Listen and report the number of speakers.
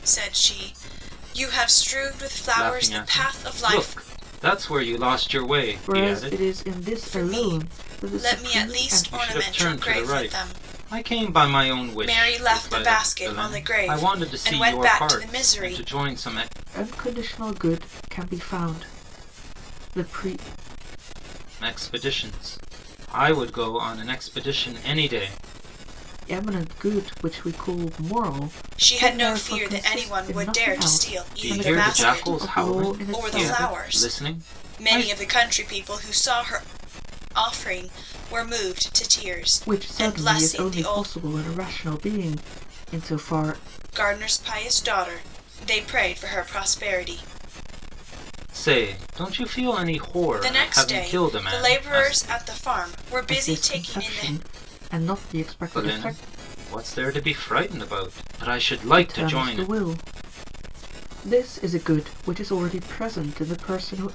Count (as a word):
three